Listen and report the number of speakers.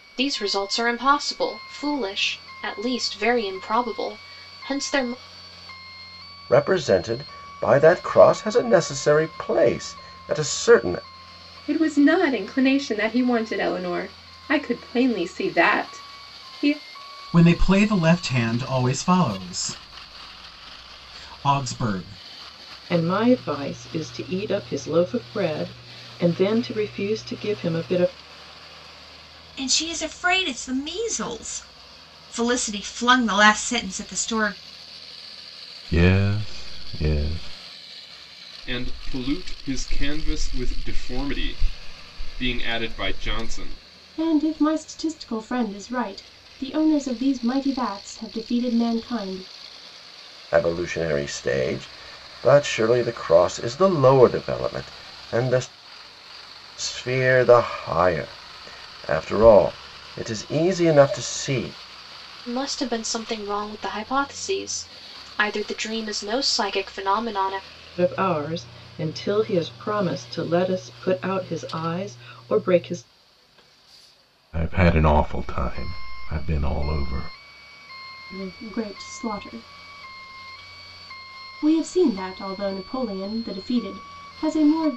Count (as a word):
nine